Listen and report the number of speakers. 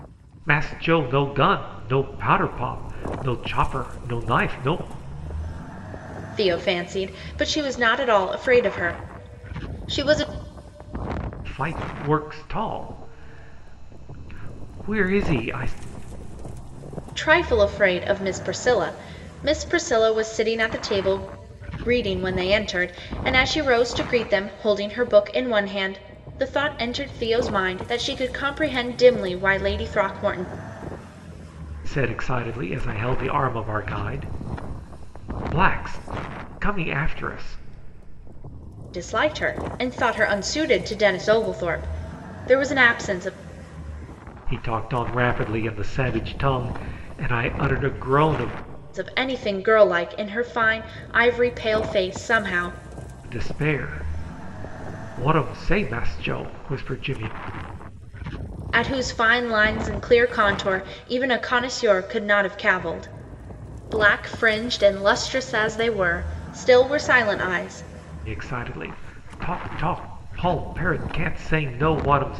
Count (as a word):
two